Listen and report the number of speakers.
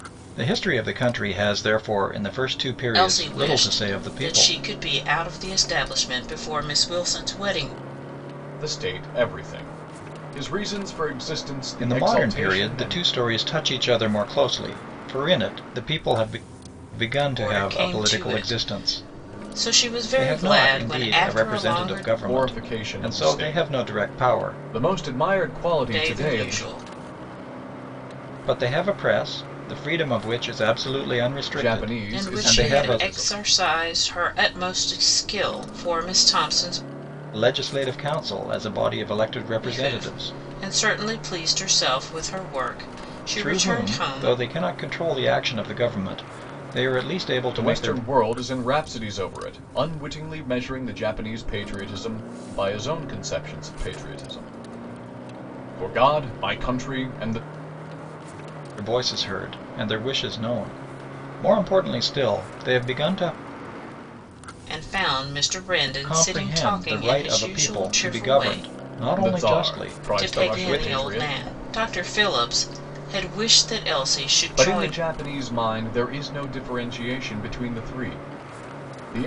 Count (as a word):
three